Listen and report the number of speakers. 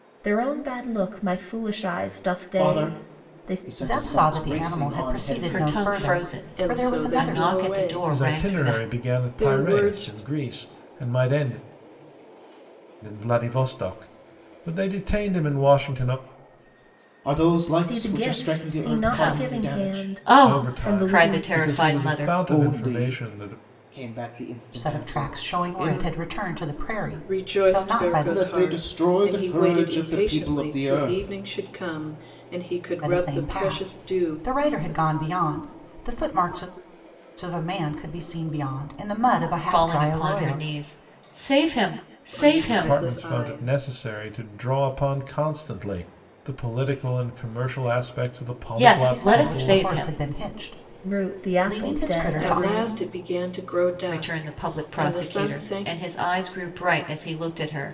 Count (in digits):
6